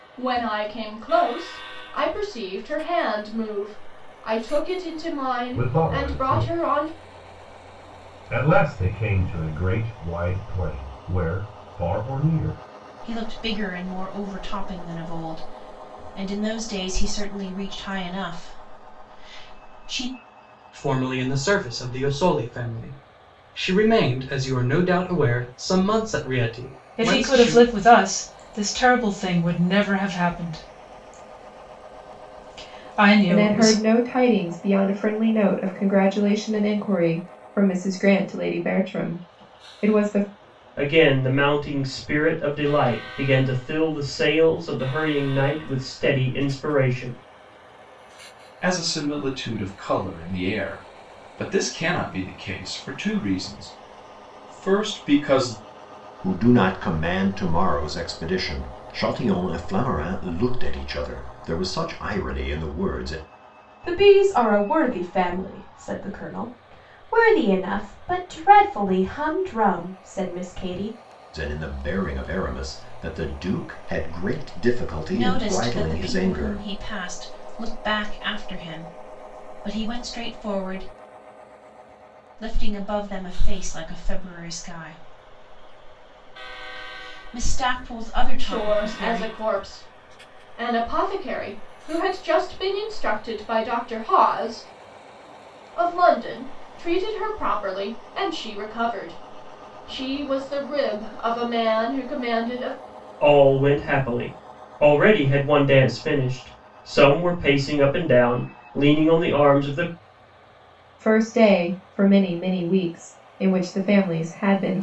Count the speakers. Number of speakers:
ten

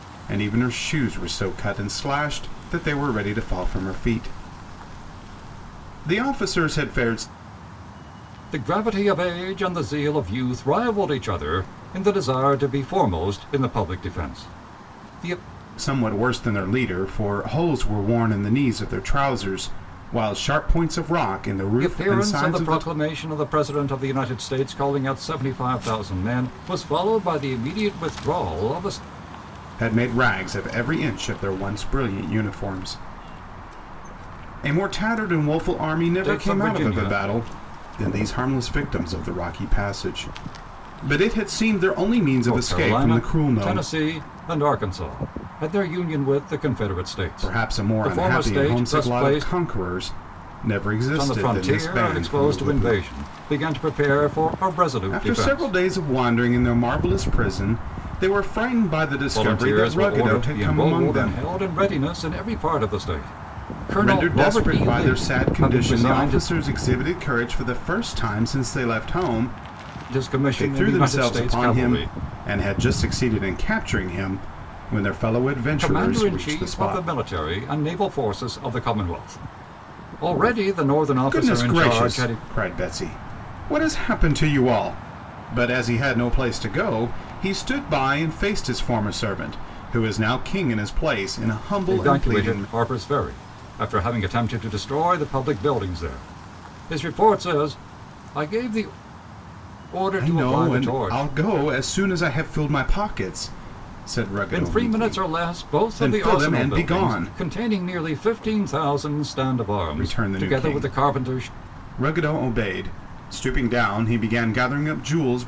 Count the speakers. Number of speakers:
two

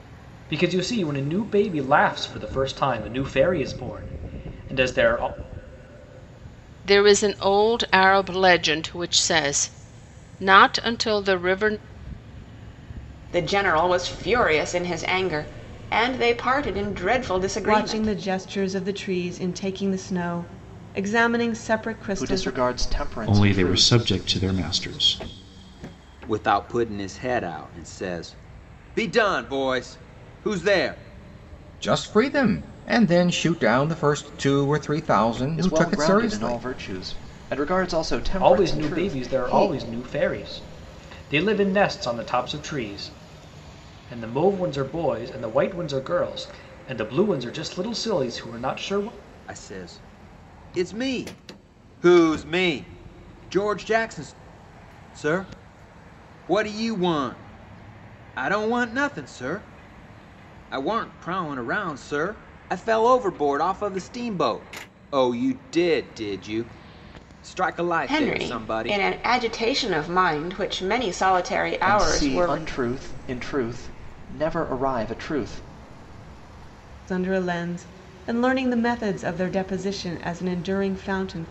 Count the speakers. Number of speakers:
eight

